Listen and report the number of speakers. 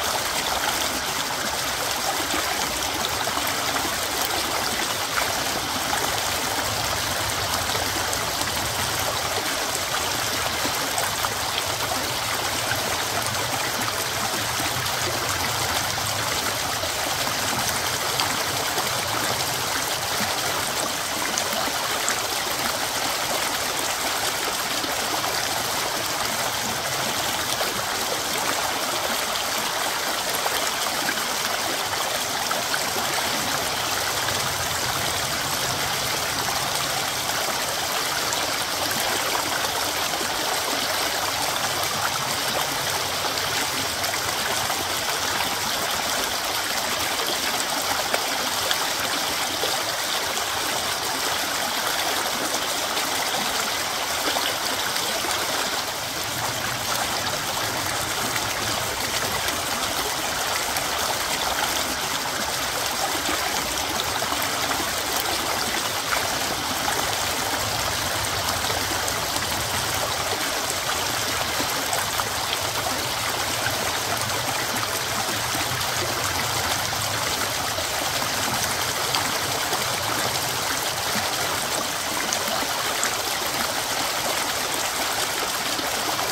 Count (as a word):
zero